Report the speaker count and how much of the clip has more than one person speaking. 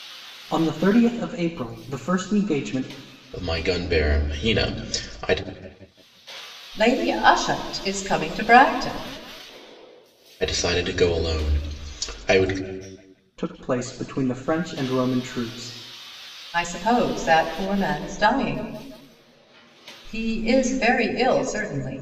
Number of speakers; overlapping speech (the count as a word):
three, no overlap